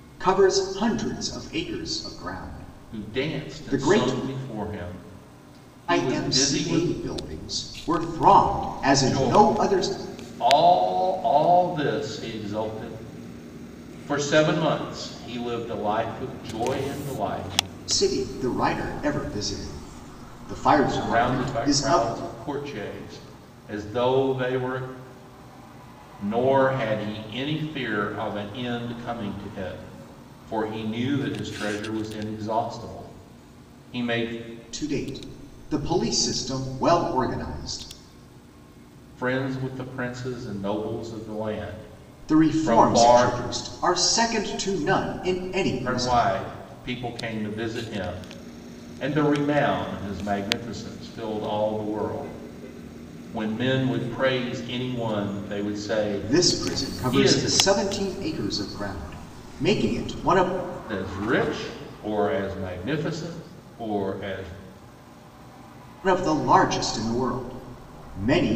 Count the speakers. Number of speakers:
2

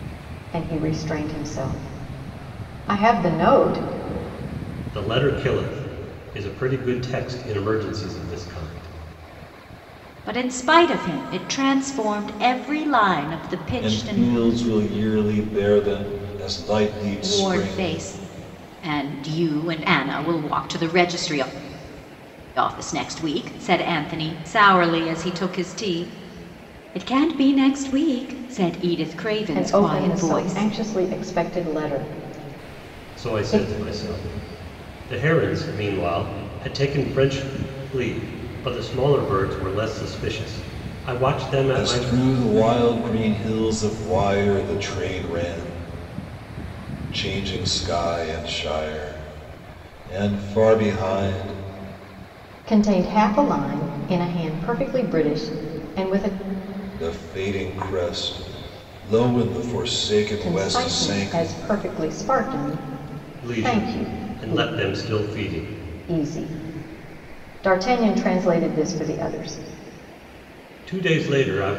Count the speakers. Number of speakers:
4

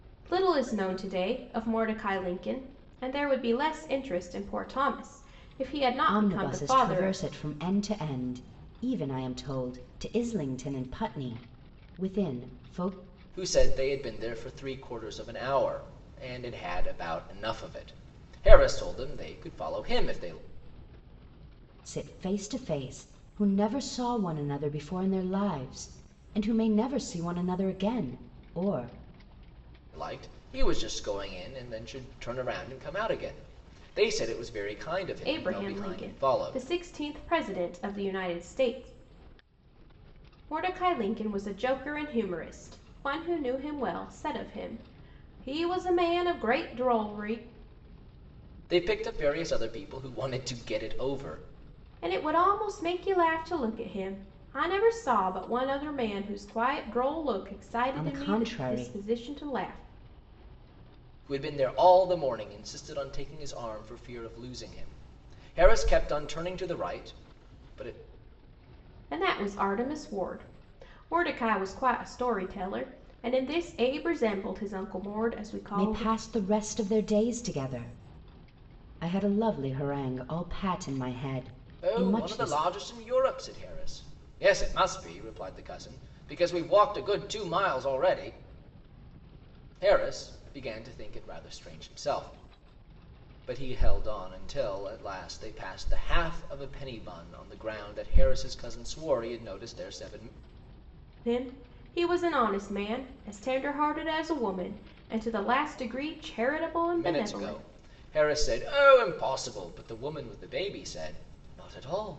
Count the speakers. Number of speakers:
3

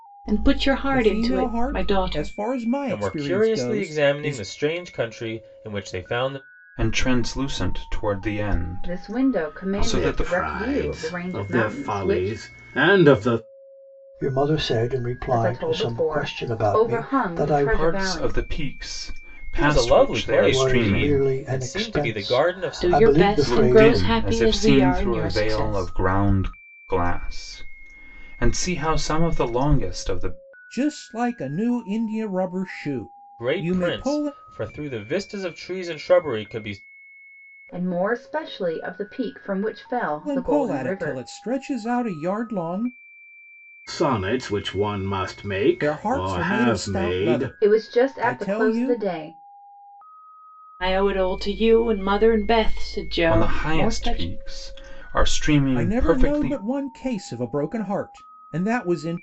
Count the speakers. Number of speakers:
7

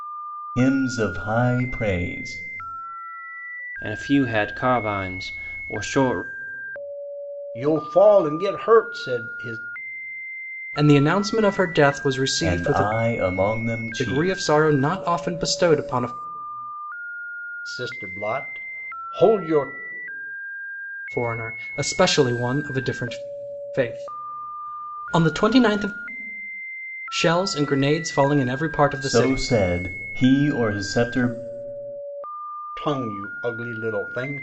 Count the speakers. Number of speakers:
4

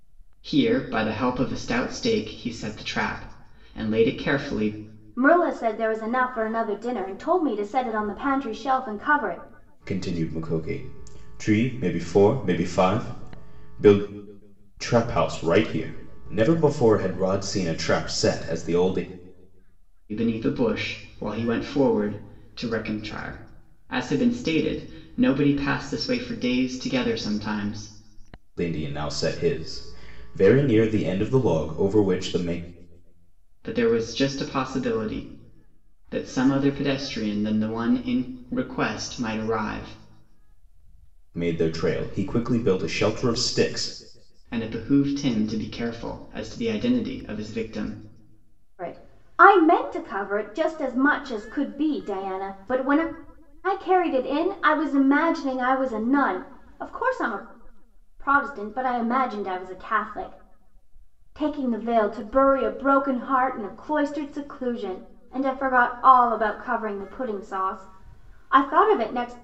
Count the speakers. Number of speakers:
3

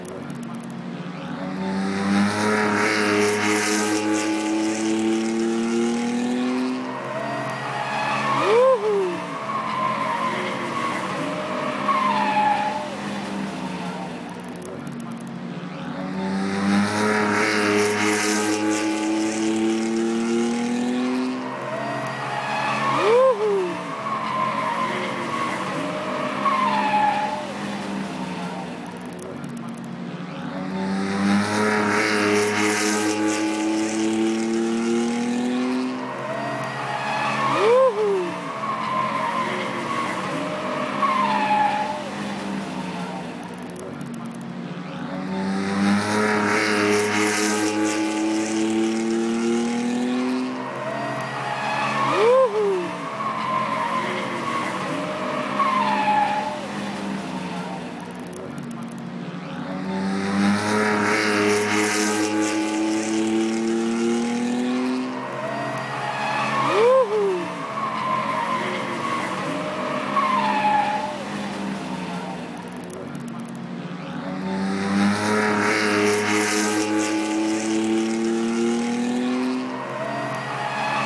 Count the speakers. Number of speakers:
0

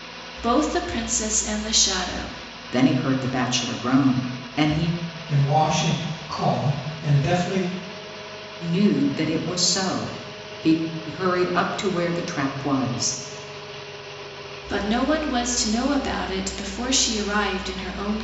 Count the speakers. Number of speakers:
3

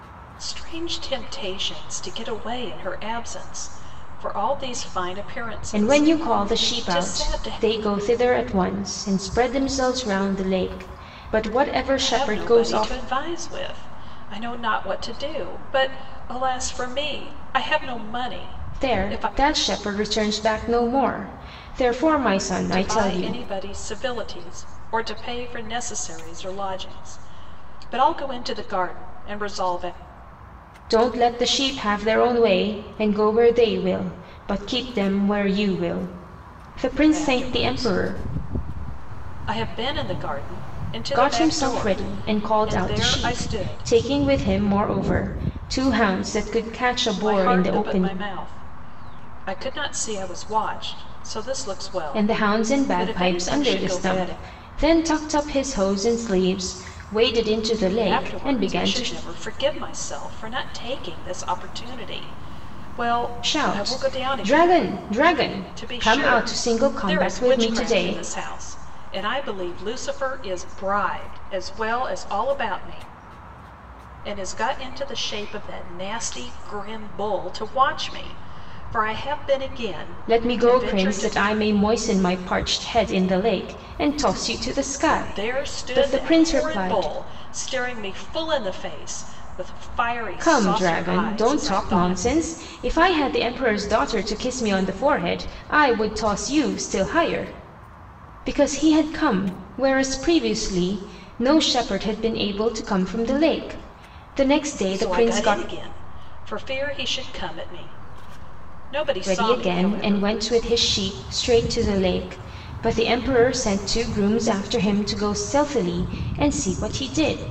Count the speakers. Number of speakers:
2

